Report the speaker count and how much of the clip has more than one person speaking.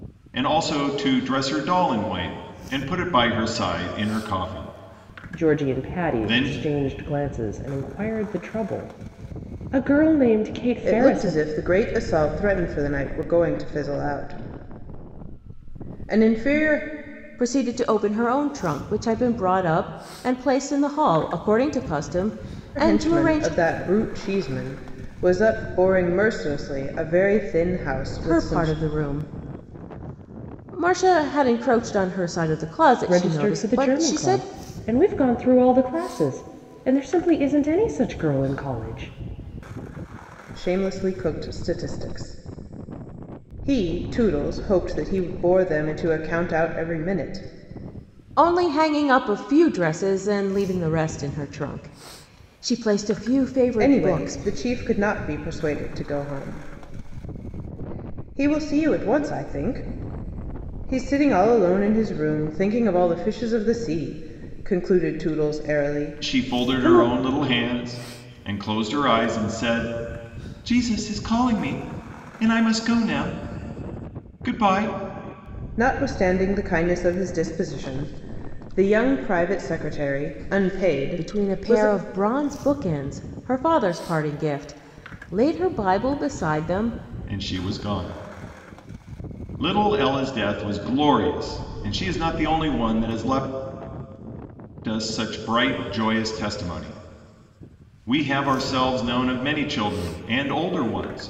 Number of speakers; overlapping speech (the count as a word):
four, about 7%